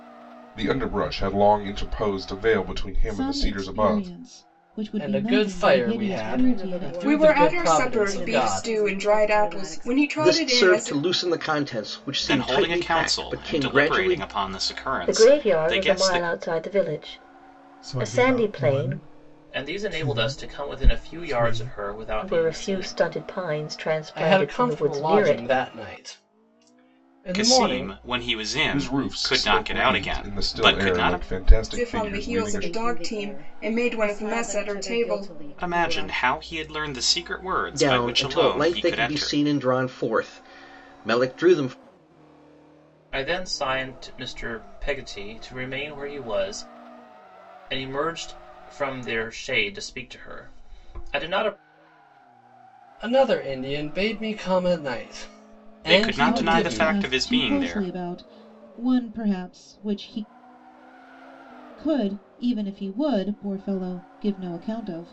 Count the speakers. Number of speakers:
10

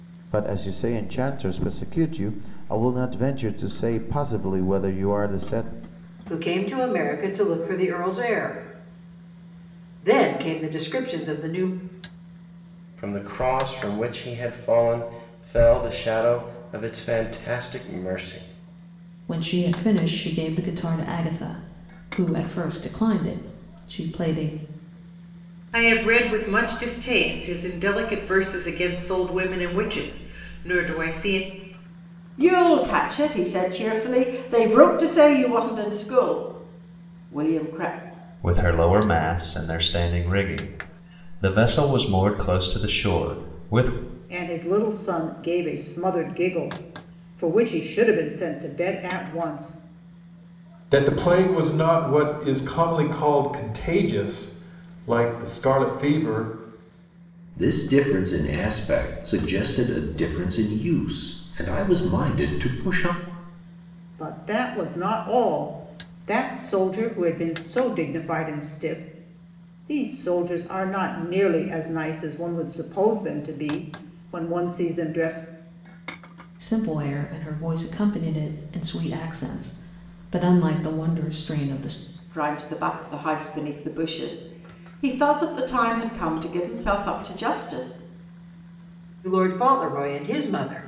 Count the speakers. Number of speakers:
10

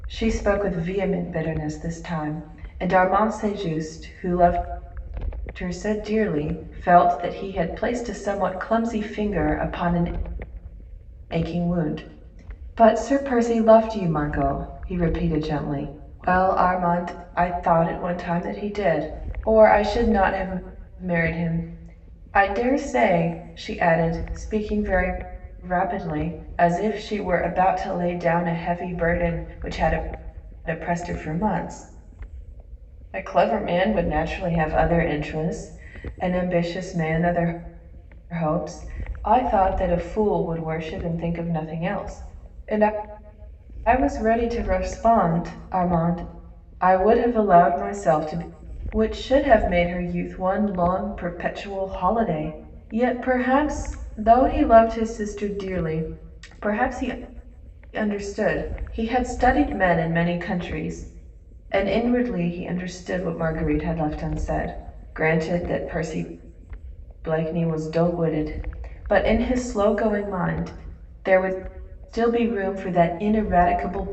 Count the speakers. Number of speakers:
1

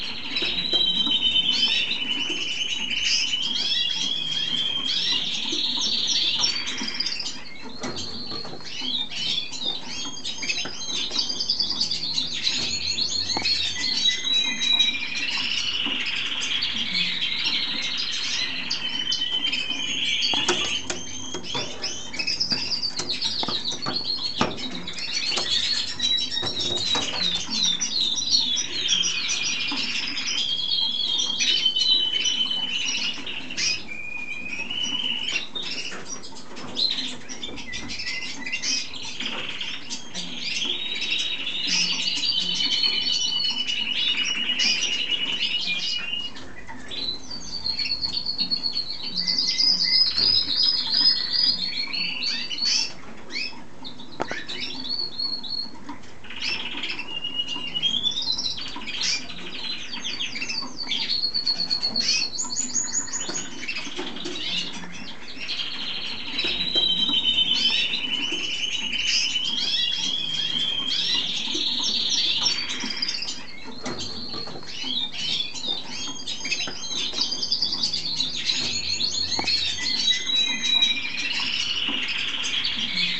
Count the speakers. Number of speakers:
0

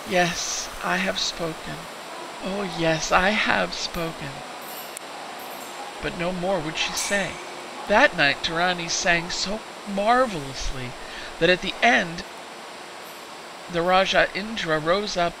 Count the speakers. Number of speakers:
1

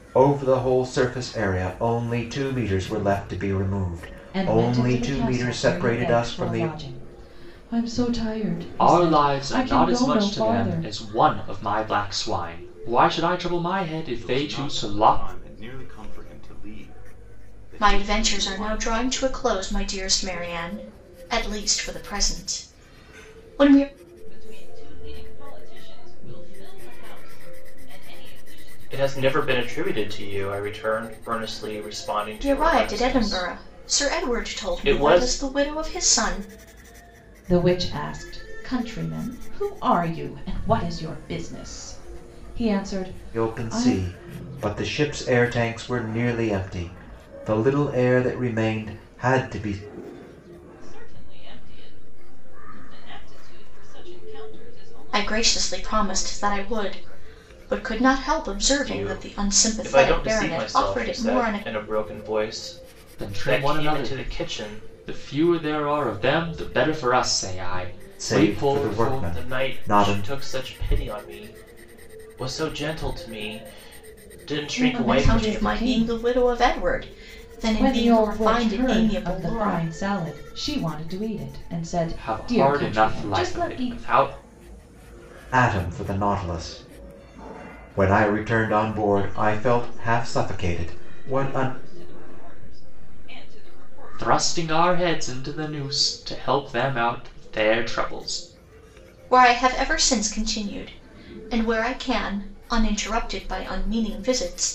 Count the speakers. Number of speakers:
7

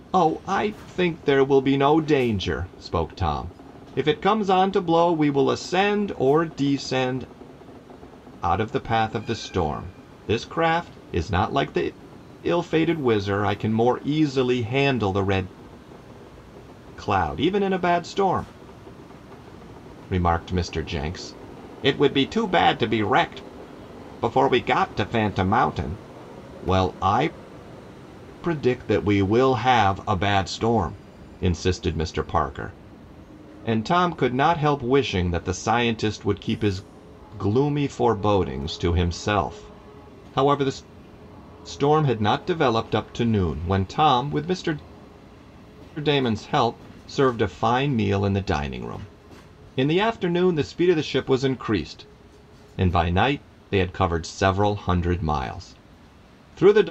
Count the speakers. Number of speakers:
1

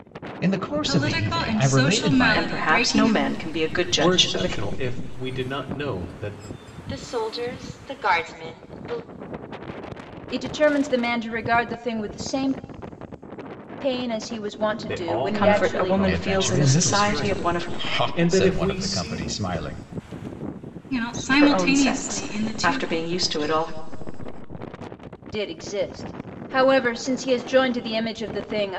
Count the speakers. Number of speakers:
6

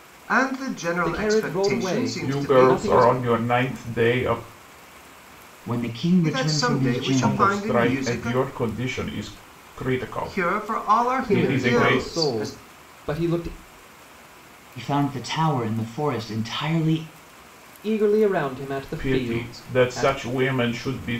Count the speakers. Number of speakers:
4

